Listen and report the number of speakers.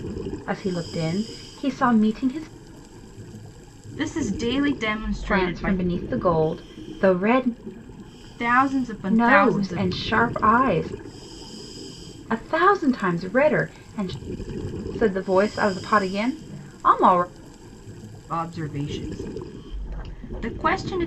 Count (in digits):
2